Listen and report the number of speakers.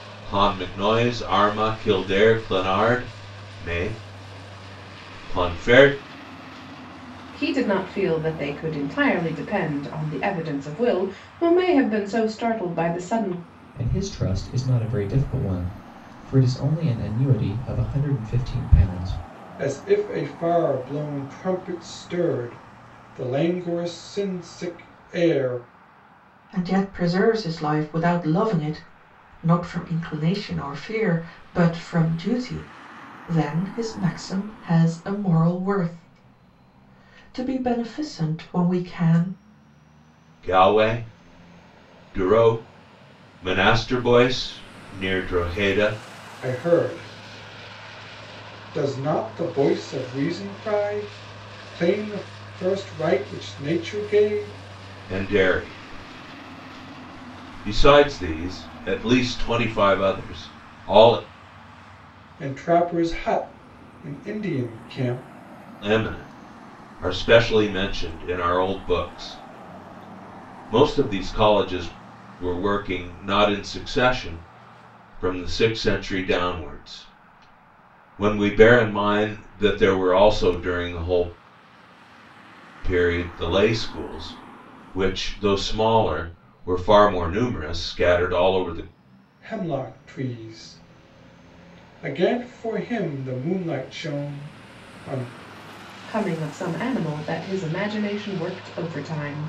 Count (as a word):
five